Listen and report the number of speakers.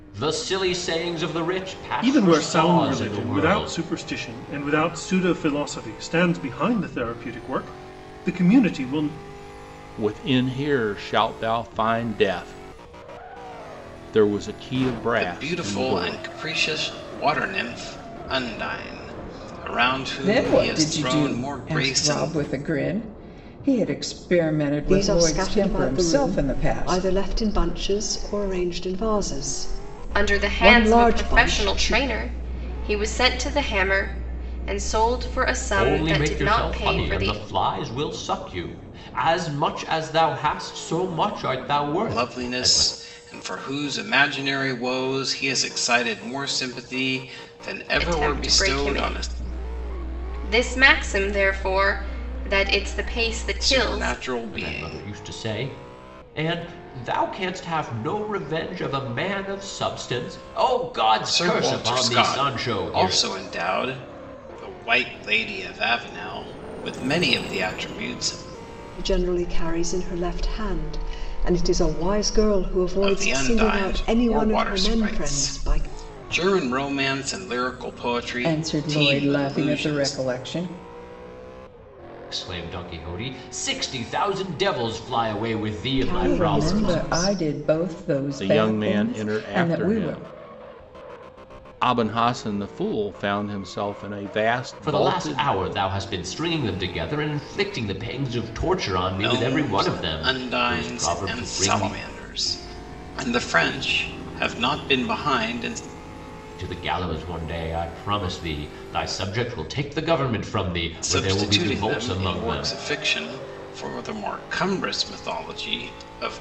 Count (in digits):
7